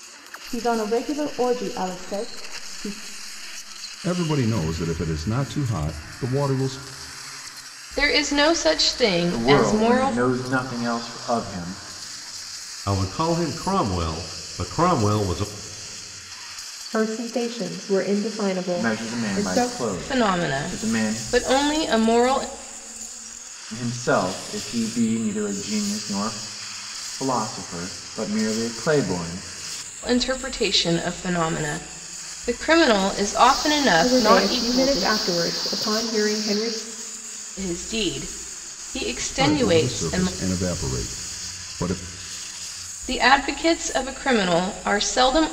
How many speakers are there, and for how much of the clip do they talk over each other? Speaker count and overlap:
6, about 12%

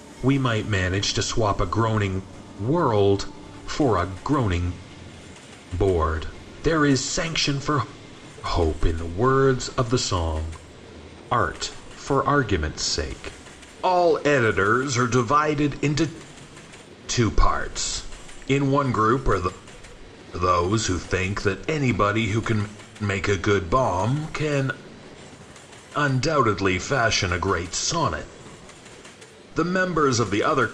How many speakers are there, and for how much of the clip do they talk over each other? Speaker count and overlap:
1, no overlap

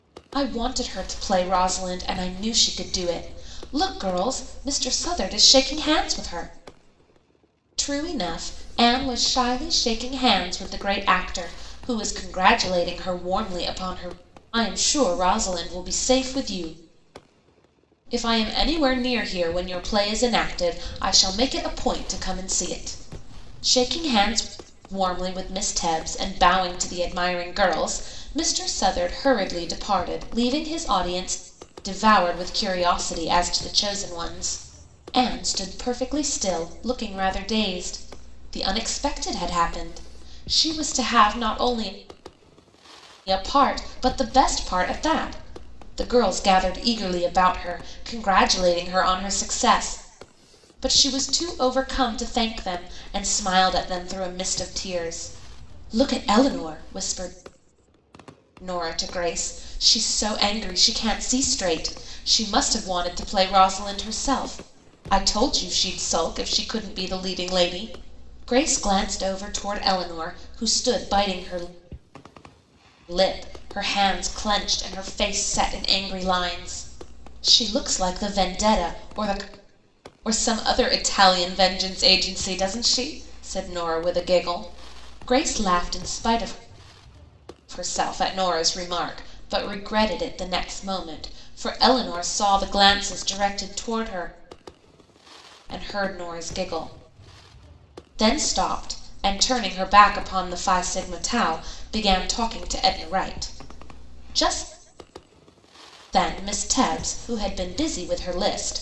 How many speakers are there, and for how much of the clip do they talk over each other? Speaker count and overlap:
1, no overlap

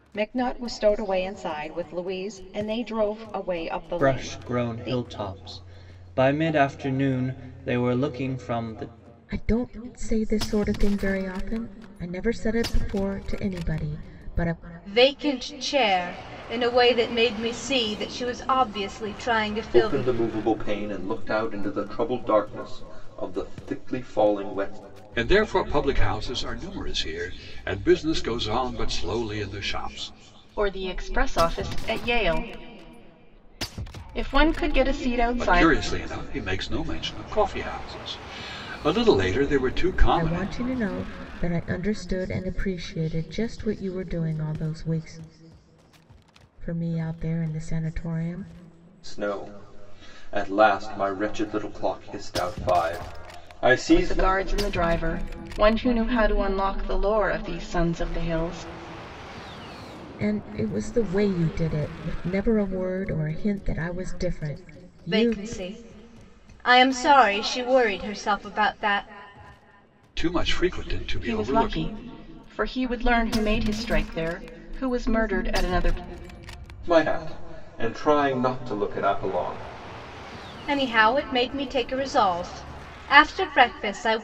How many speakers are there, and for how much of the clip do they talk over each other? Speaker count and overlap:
7, about 5%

